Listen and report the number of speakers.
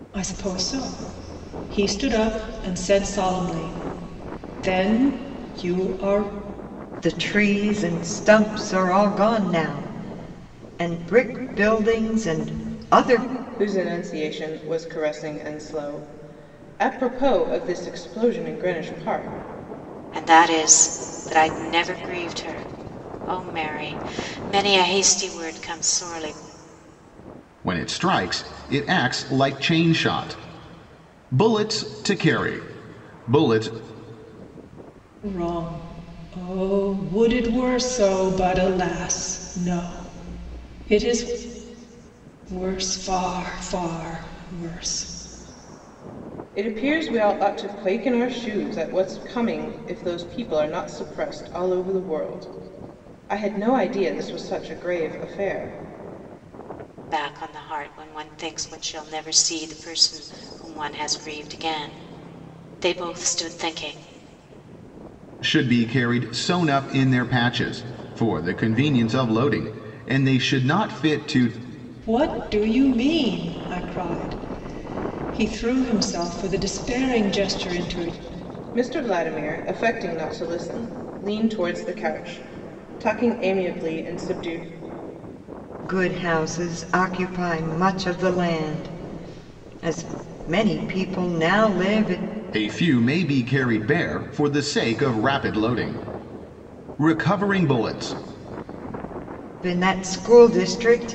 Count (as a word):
five